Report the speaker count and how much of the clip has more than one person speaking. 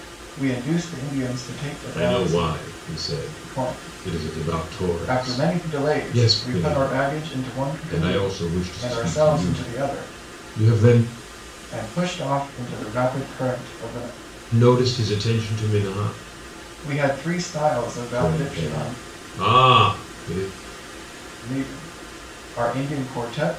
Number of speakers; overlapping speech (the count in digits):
2, about 34%